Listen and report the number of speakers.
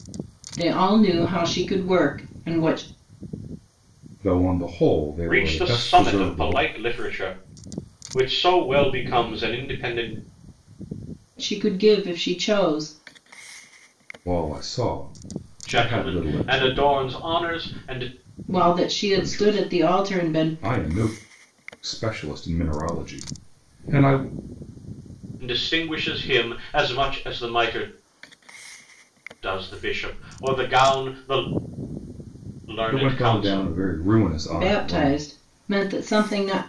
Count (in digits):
3